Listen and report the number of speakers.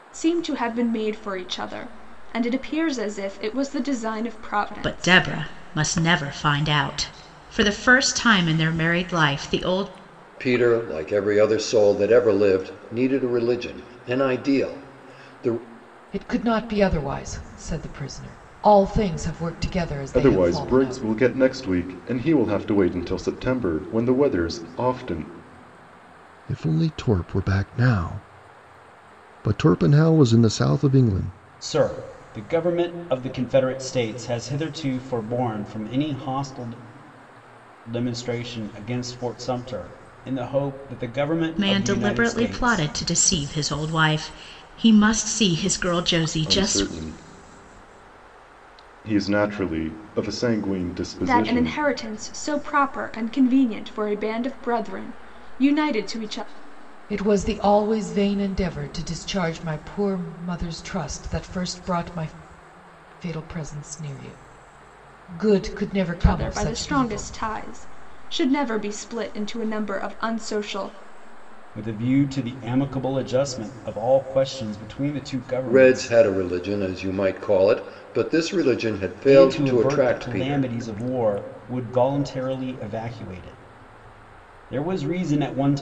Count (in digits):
7